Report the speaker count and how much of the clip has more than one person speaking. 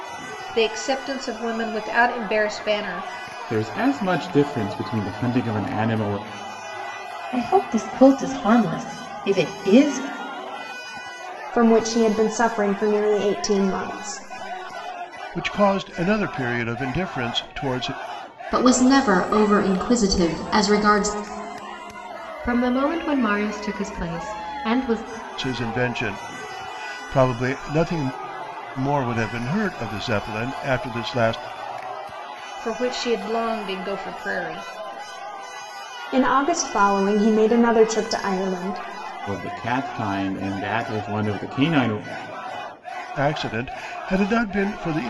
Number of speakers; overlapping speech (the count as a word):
seven, no overlap